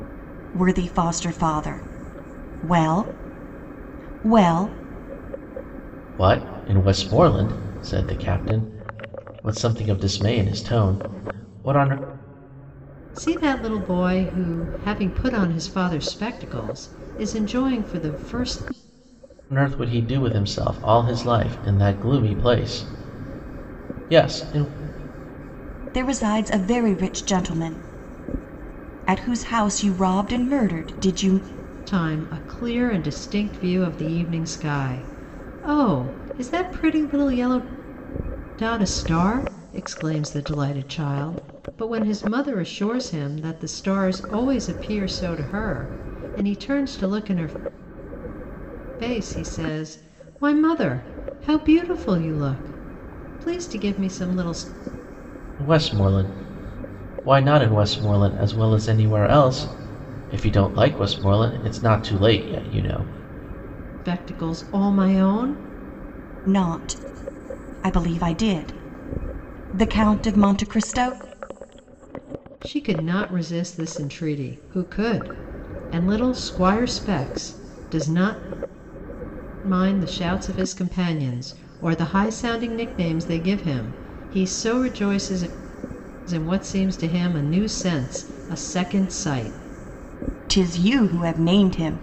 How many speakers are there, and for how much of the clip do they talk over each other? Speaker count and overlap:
3, no overlap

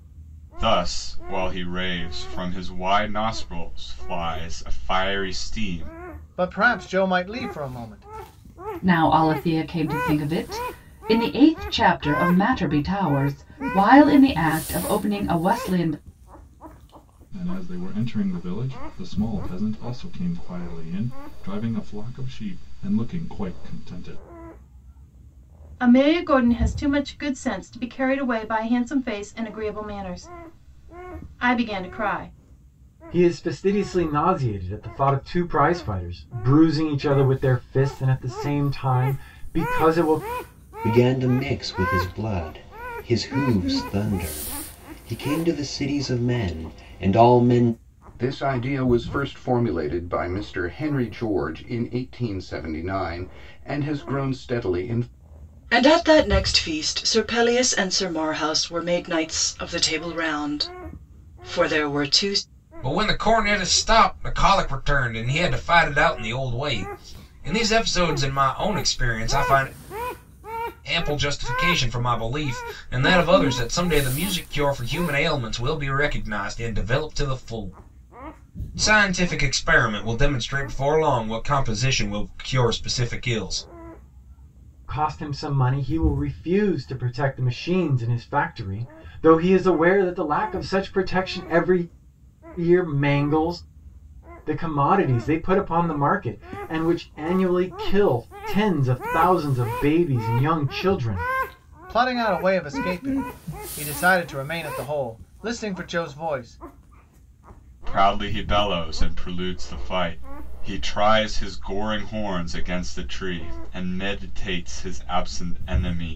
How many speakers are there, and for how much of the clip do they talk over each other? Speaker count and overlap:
10, no overlap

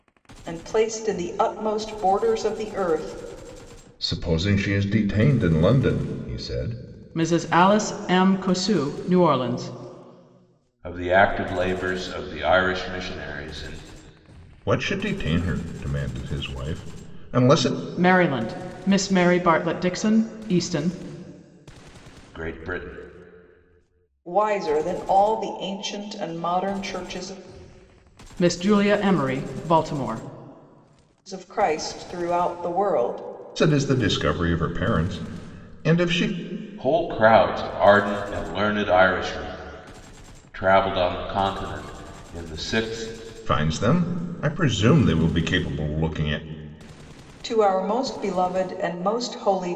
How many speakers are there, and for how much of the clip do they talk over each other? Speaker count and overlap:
4, no overlap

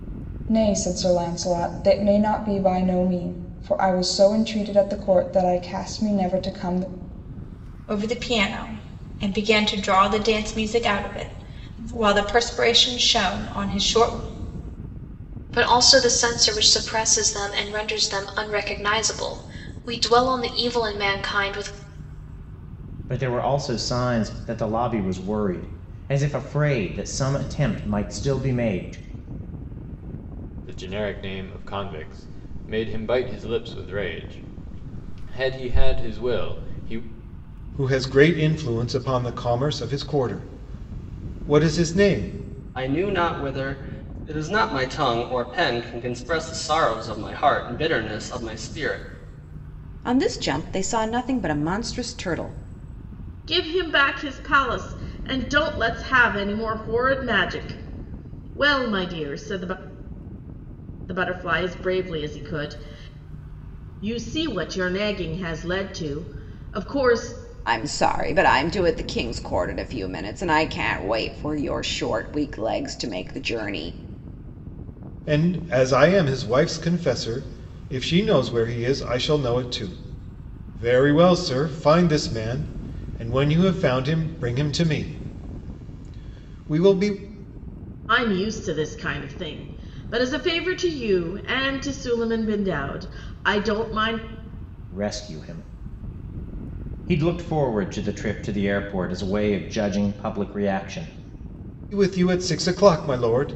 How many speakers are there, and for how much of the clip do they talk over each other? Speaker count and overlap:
9, no overlap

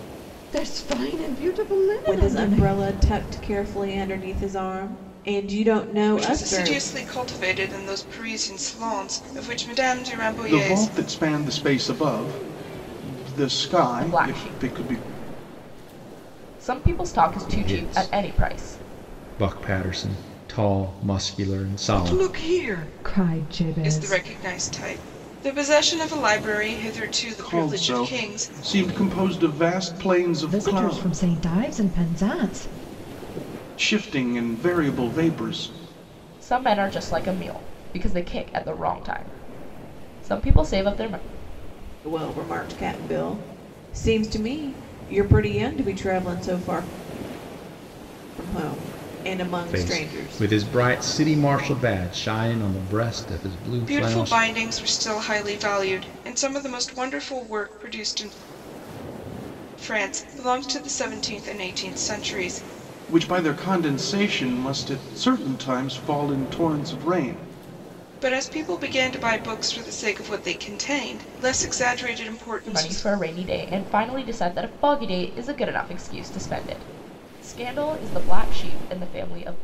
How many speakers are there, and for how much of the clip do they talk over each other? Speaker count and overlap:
6, about 12%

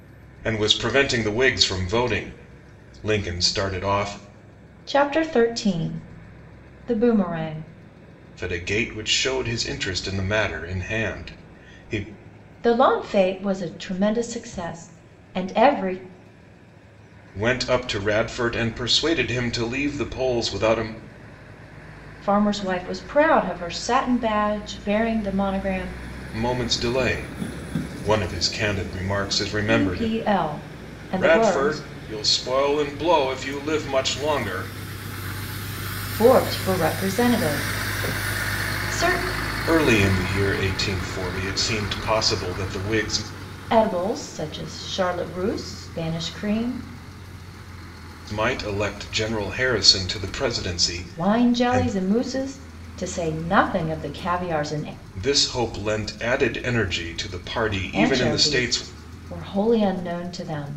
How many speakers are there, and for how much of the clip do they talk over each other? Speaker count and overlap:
2, about 5%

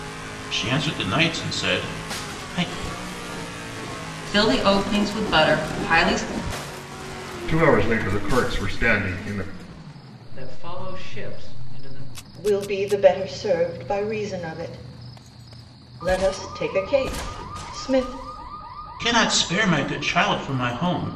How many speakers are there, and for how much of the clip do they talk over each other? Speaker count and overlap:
5, no overlap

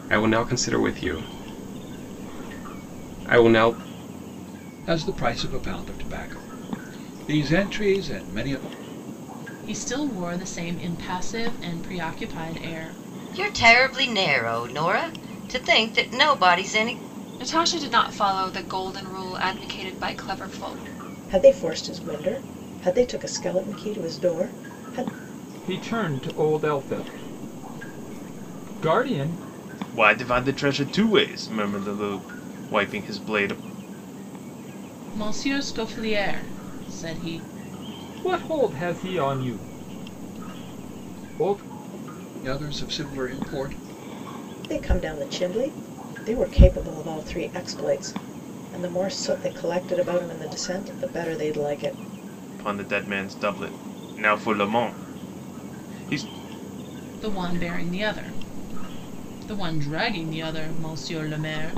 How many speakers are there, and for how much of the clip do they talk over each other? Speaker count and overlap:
8, no overlap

